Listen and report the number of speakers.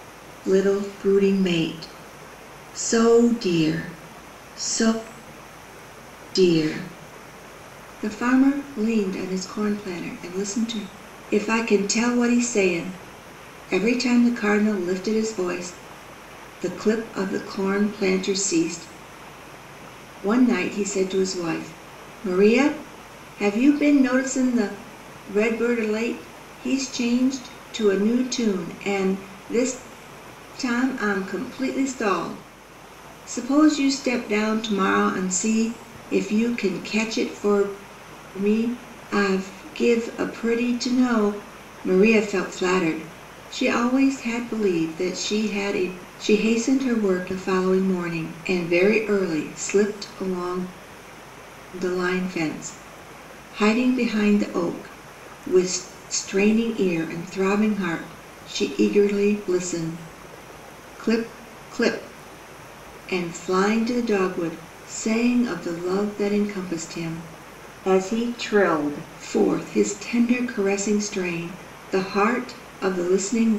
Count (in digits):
1